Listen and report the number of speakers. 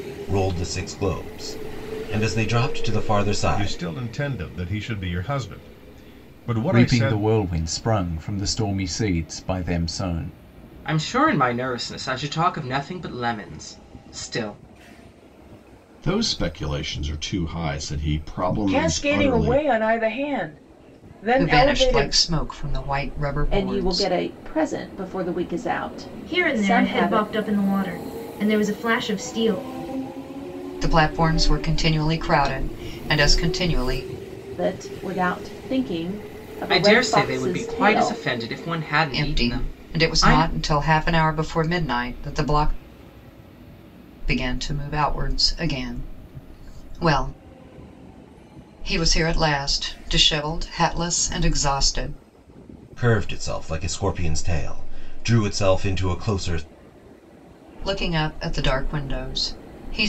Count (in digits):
9